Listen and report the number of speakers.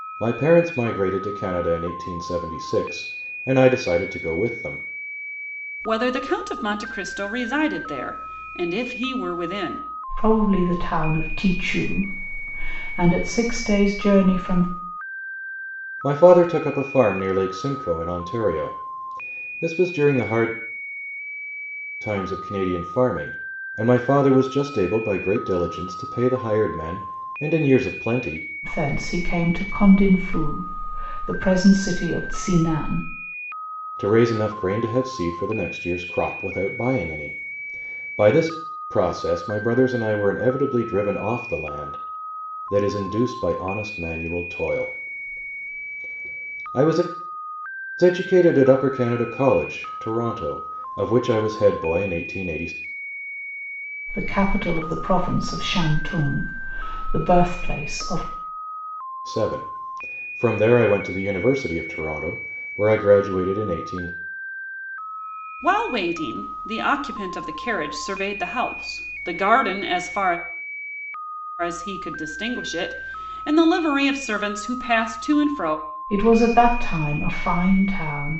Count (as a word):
three